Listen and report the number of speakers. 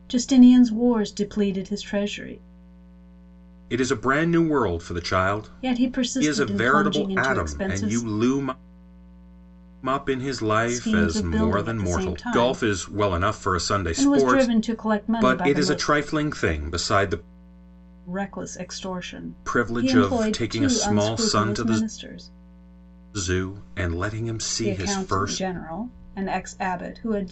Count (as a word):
two